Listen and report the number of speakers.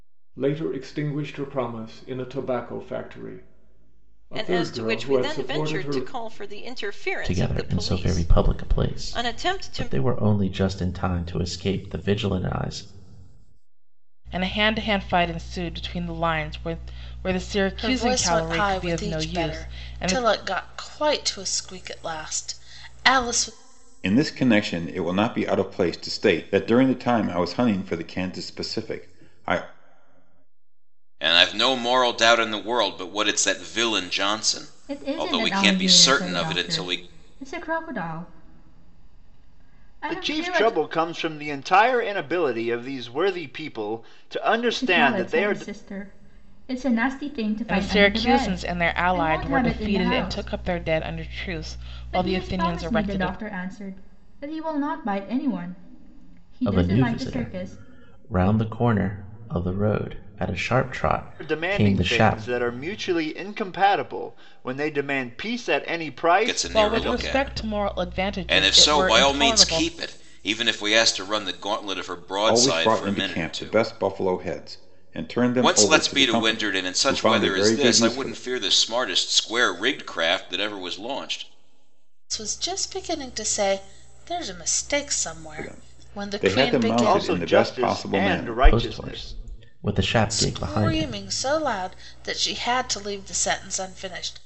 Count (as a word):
nine